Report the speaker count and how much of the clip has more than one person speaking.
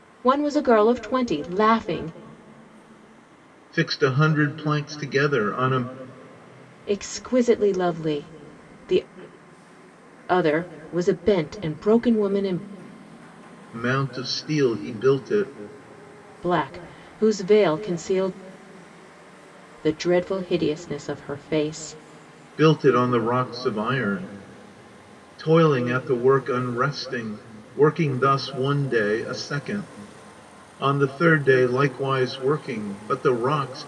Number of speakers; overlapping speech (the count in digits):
2, no overlap